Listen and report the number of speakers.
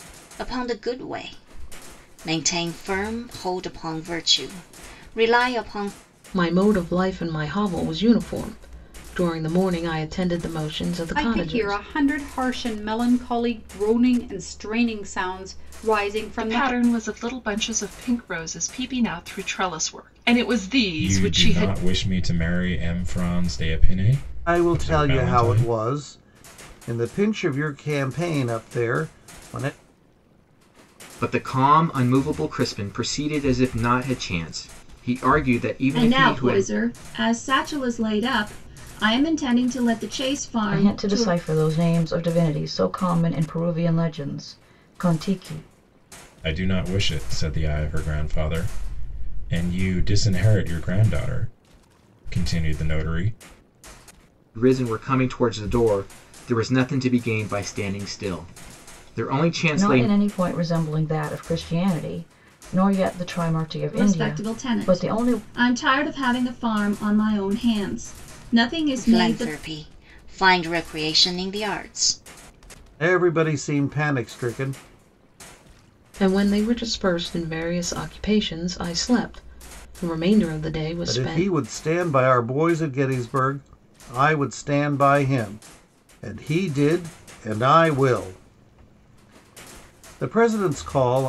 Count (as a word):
nine